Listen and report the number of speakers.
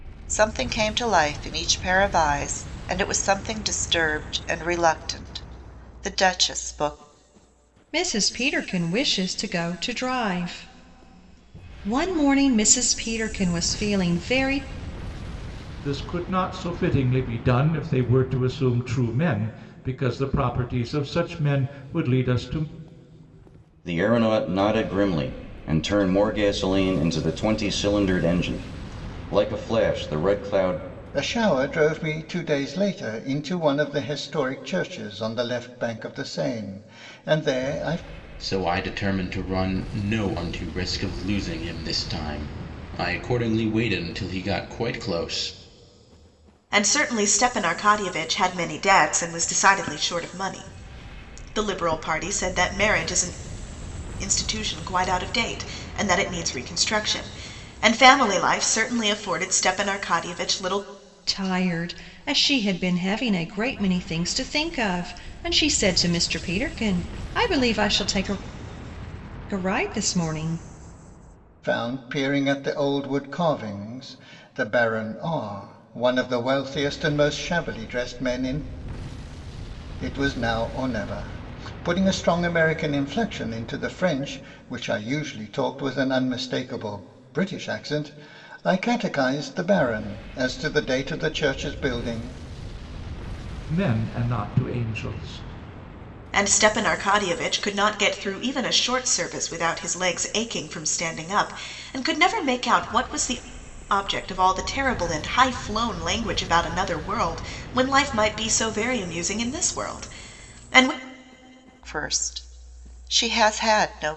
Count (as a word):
seven